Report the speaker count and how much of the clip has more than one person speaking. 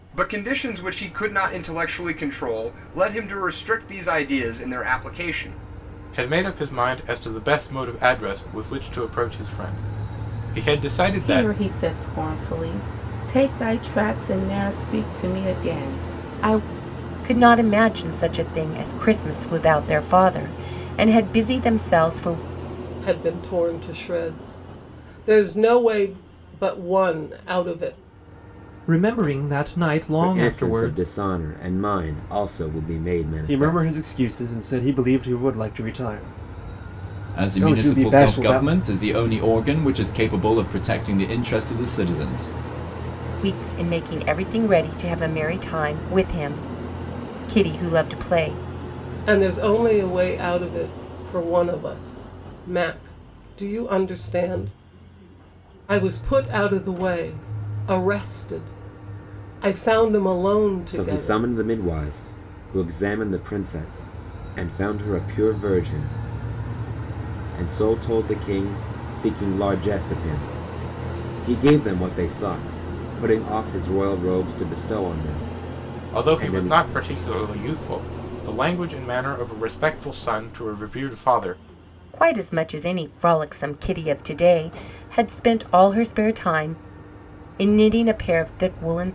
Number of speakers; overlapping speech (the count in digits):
9, about 5%